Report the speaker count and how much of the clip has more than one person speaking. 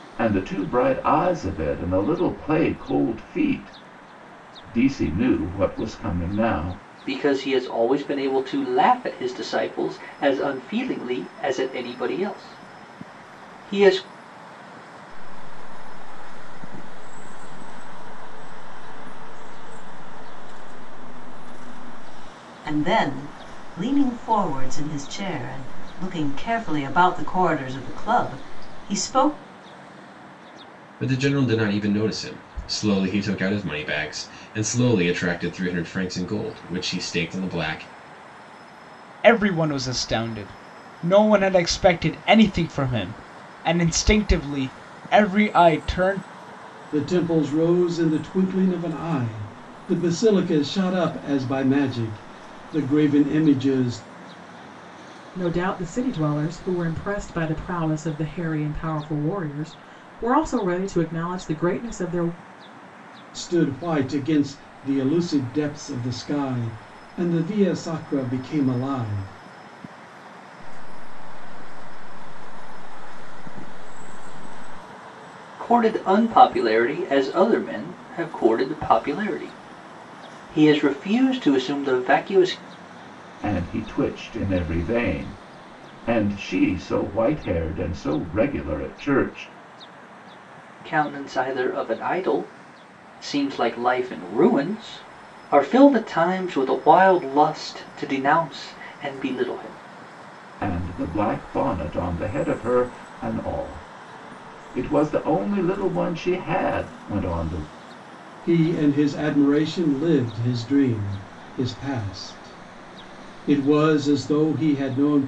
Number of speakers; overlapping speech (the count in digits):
8, no overlap